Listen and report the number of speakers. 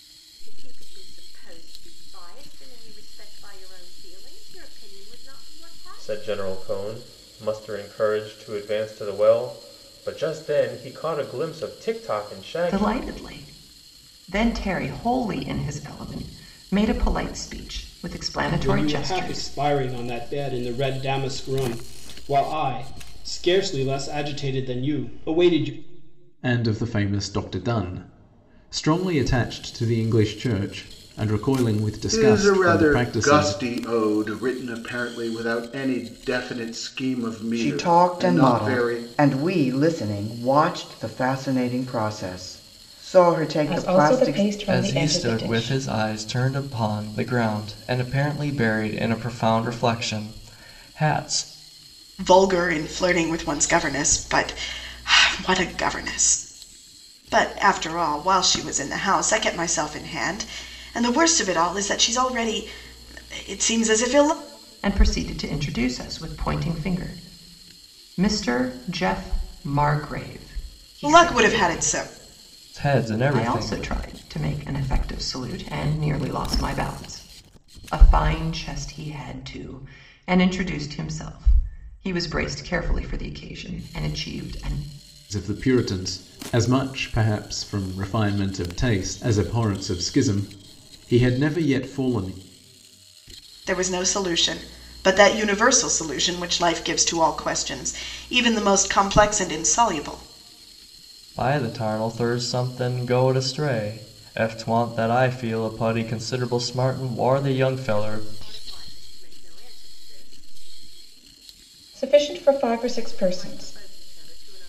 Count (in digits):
10